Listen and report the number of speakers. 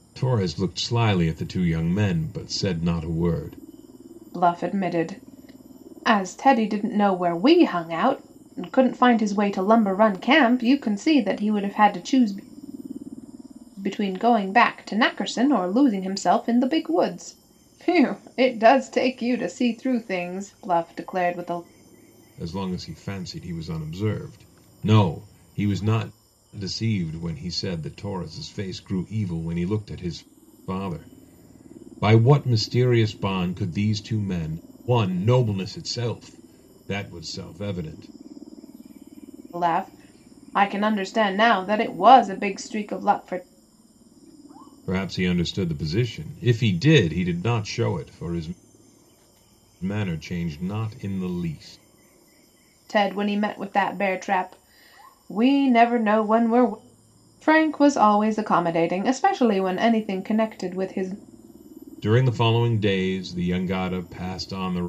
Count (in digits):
2